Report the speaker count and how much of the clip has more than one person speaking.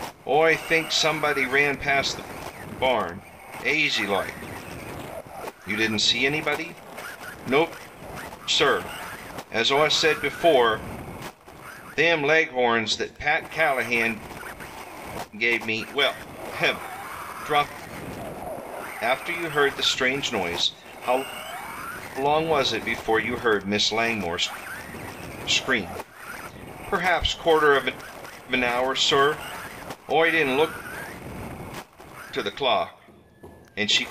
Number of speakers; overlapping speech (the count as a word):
one, no overlap